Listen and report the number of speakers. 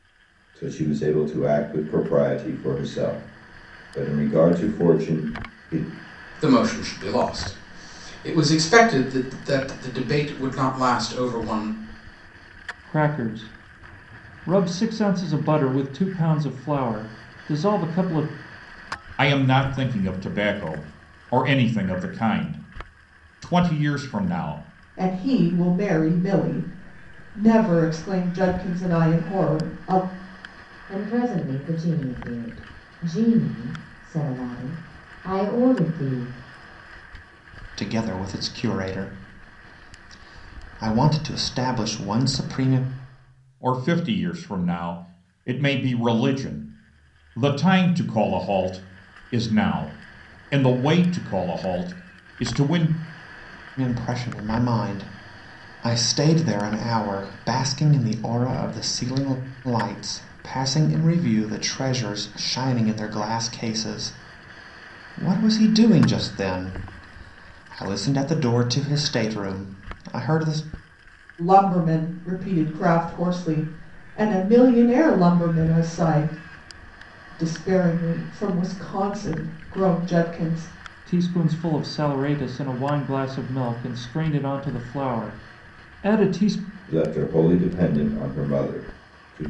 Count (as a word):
seven